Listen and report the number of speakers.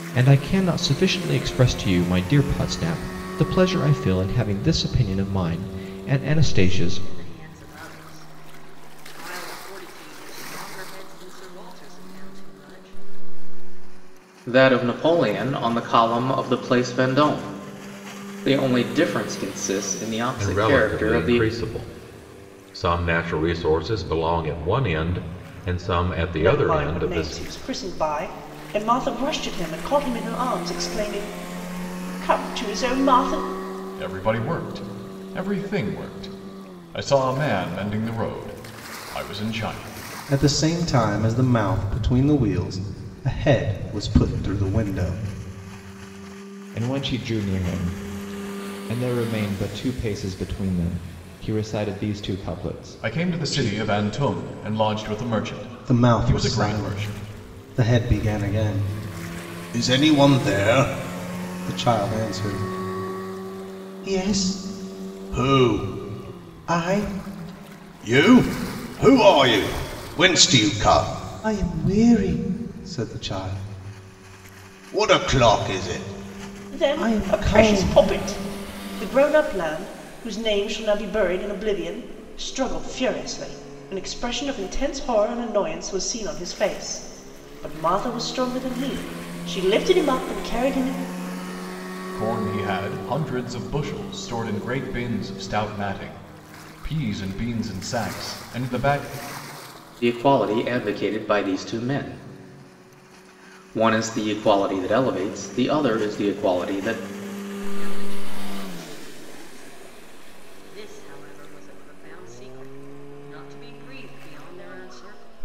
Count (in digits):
8